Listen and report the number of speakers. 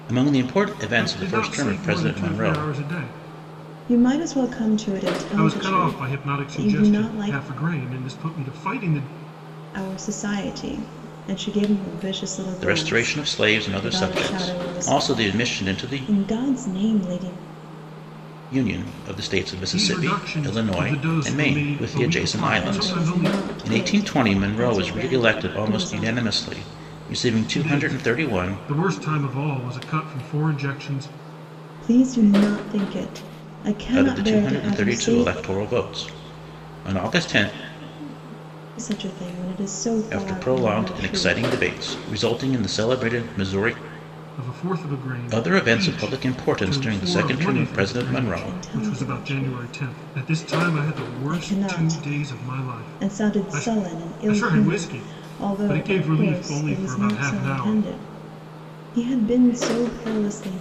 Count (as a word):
three